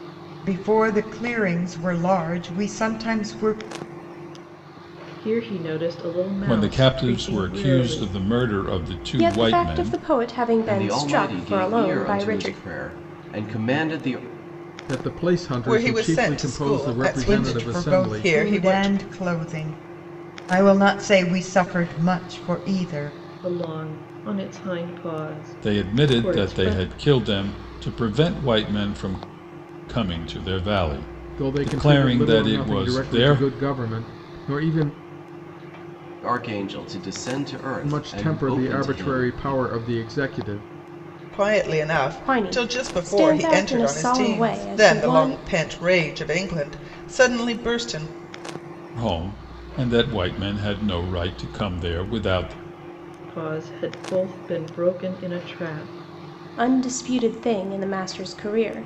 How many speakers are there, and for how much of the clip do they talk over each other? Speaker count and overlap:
seven, about 28%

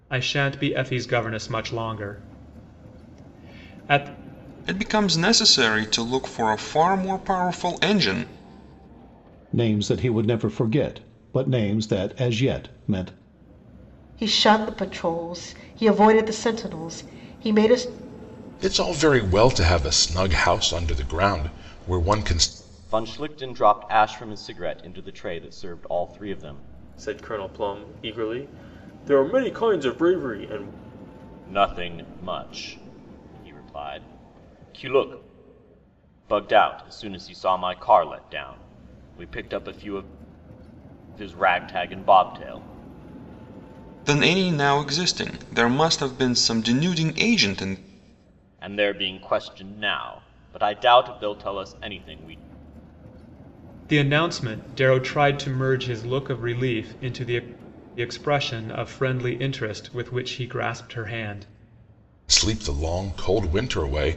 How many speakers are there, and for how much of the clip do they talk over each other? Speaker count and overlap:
seven, no overlap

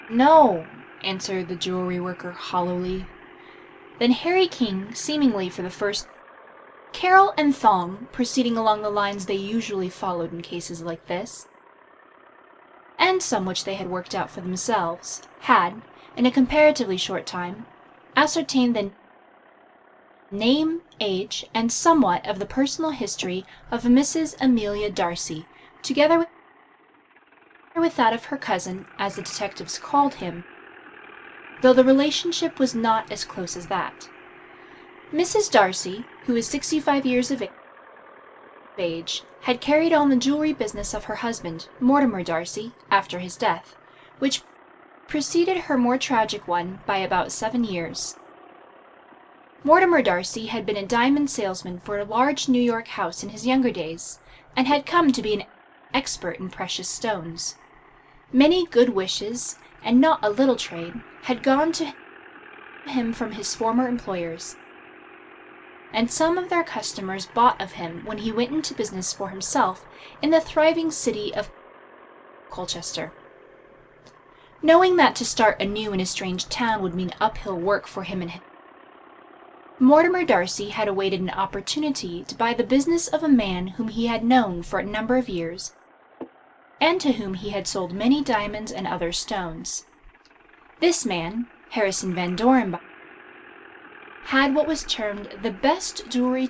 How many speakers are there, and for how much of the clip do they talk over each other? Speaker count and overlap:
one, no overlap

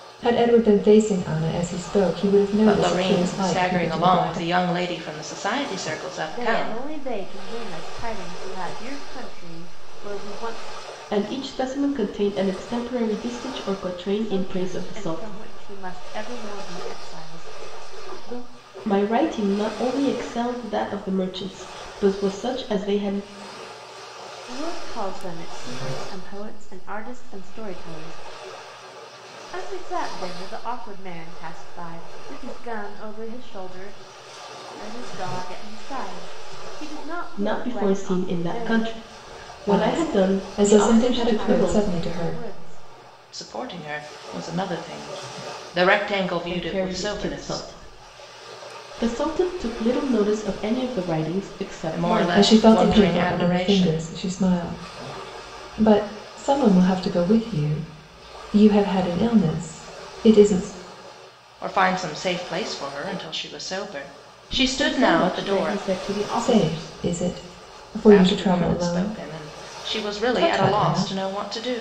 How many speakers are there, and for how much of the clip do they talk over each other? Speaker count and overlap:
four, about 22%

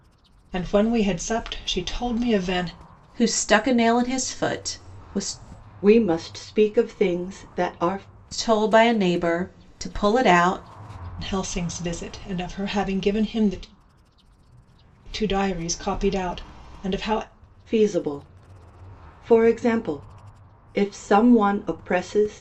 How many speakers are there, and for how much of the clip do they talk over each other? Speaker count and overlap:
three, no overlap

